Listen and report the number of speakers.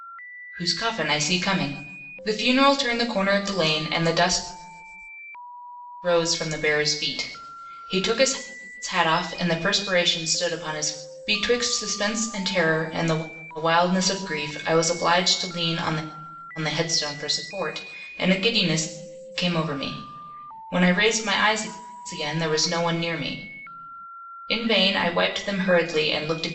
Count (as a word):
one